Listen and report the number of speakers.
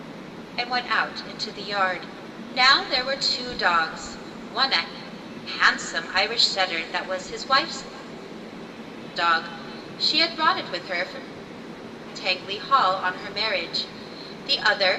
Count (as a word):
one